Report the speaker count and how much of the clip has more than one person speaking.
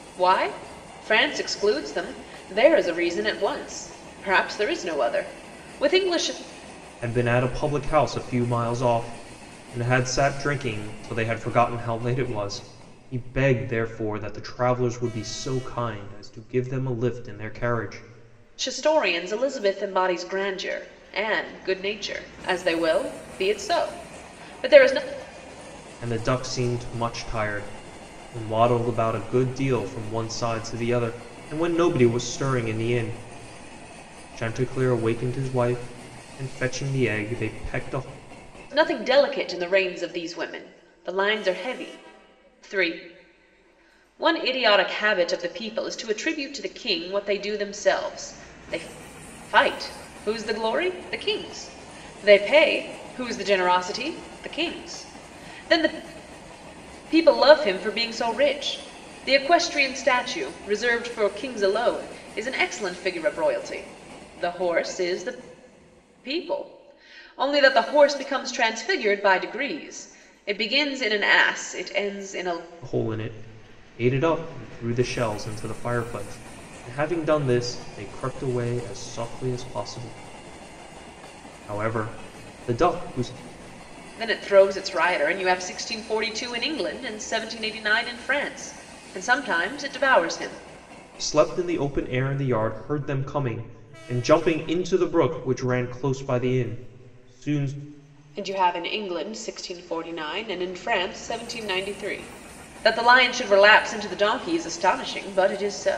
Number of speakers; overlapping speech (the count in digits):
2, no overlap